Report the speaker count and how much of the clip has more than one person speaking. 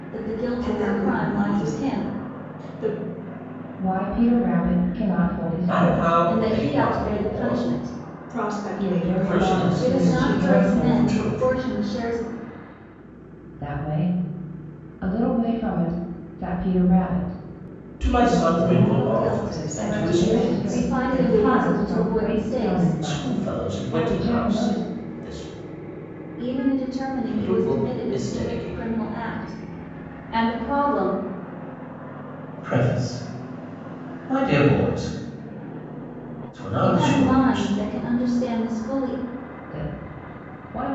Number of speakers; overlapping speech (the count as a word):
four, about 39%